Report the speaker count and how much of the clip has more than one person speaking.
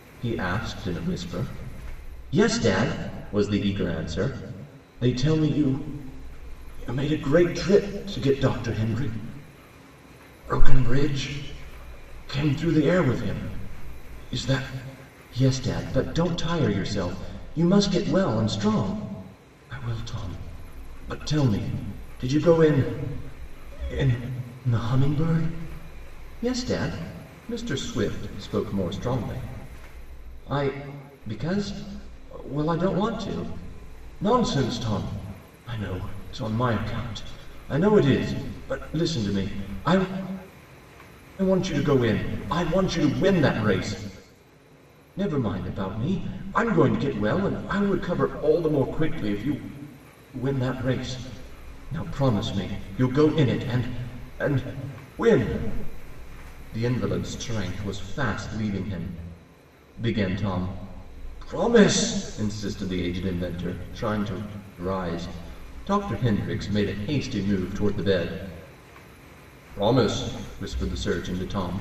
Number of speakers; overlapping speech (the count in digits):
1, no overlap